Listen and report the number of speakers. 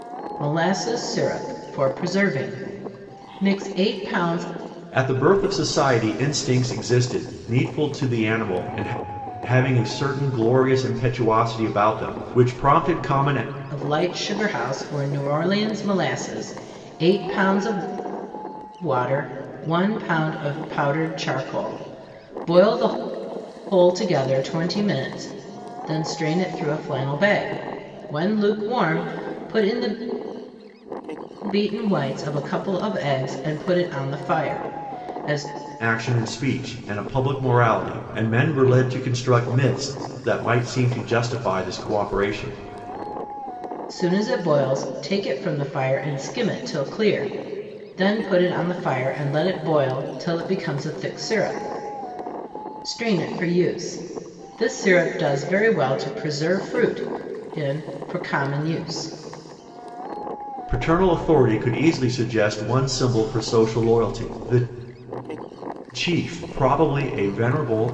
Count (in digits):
2